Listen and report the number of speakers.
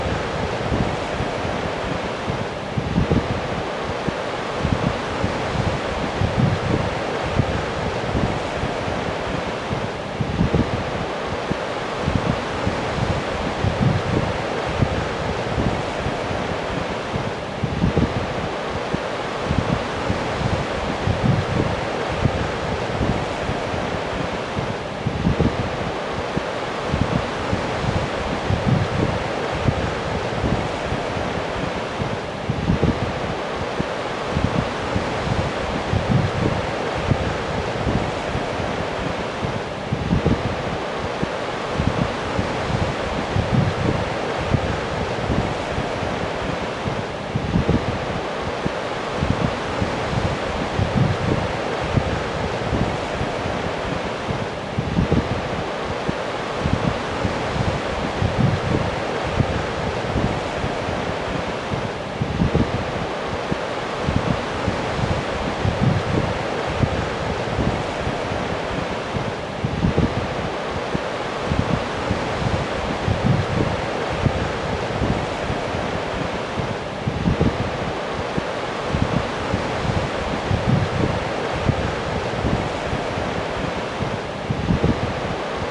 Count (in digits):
0